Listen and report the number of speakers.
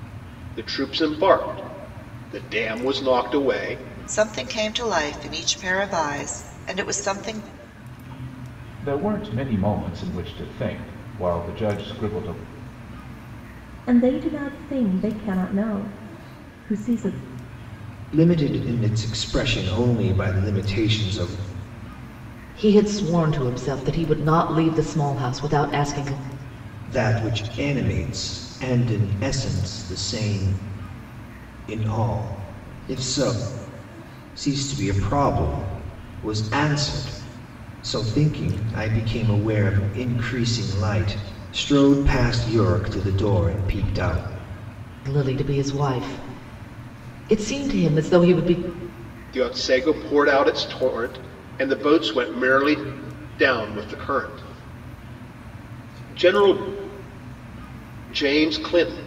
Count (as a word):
six